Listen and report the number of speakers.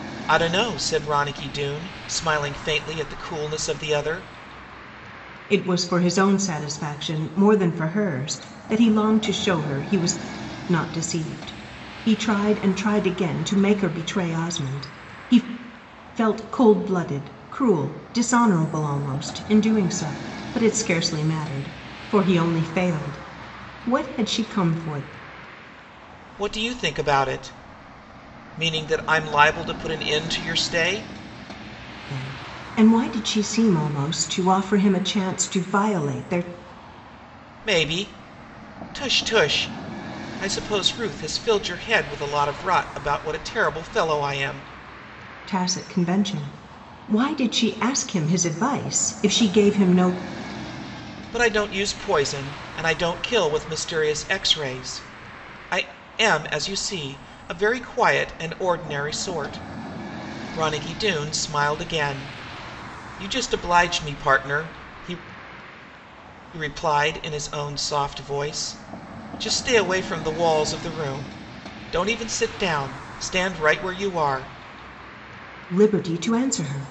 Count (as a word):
two